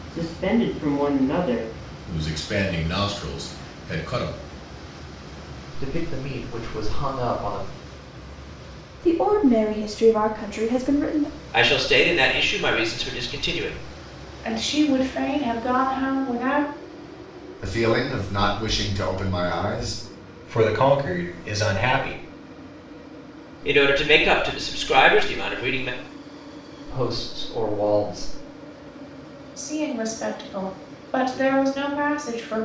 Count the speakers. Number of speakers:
eight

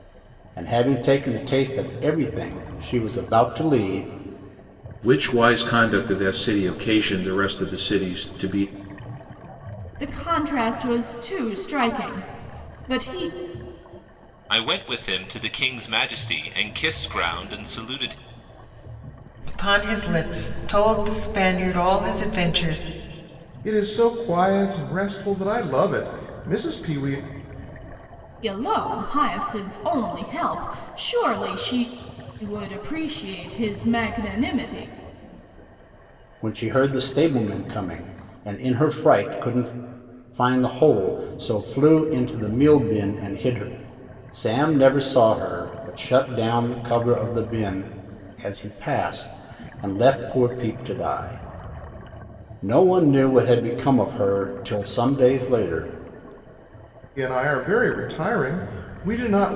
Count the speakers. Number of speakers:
six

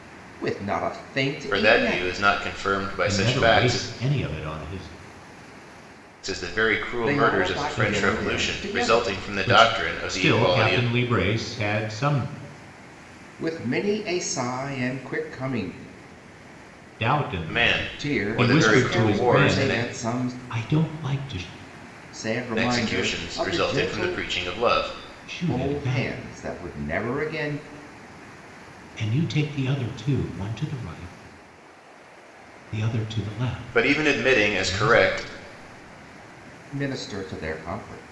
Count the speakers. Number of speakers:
three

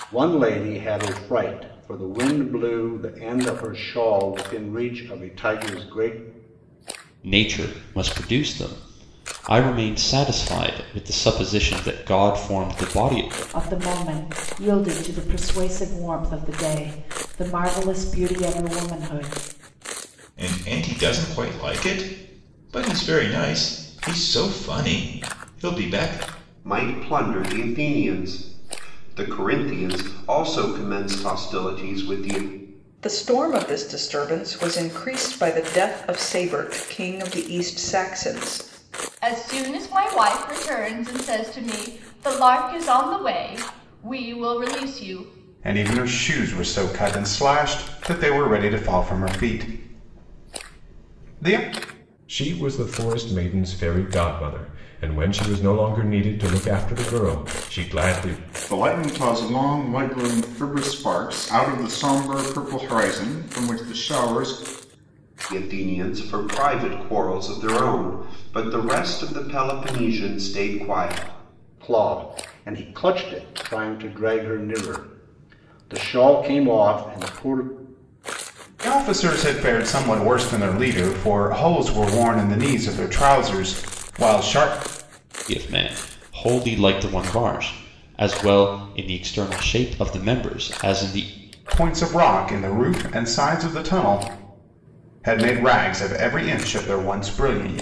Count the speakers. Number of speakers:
ten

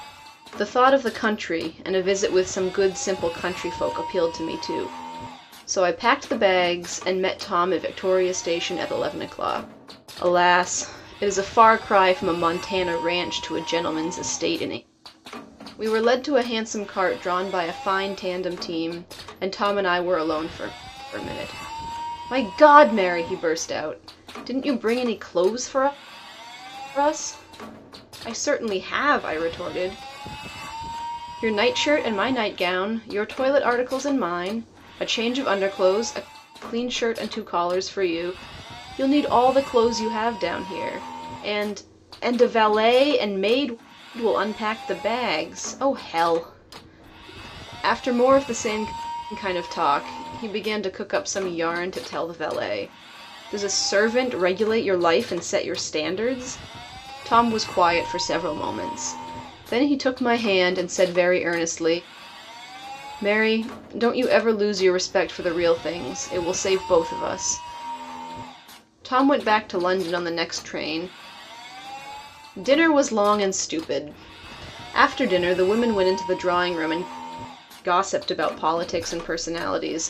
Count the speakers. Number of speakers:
one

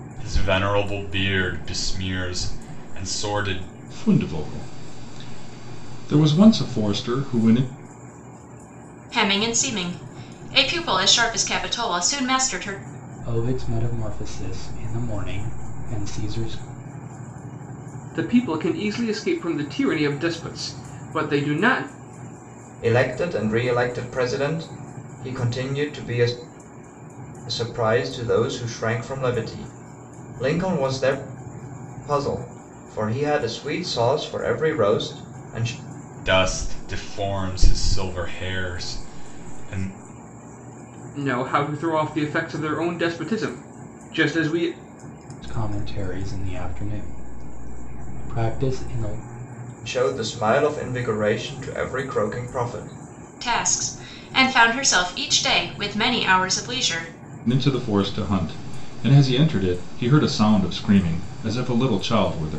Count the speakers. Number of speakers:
six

